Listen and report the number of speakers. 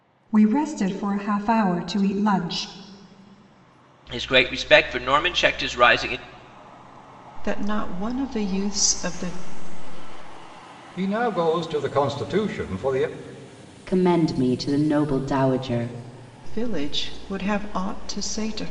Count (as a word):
five